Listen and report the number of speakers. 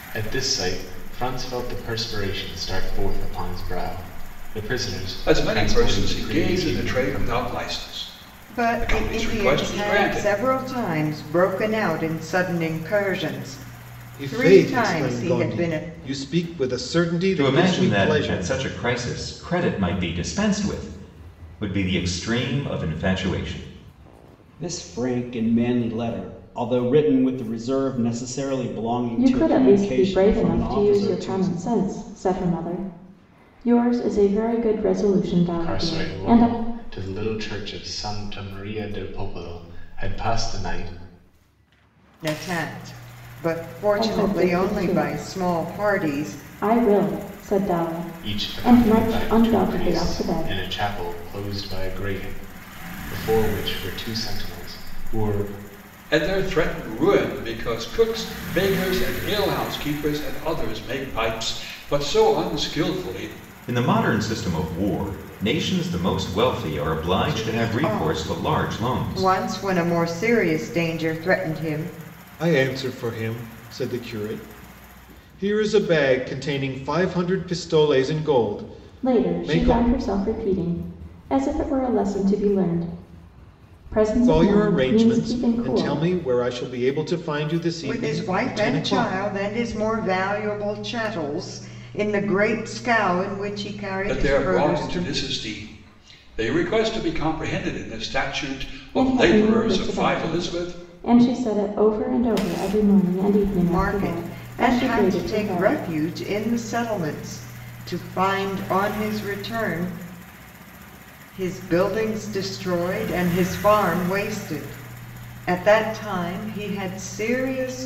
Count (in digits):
7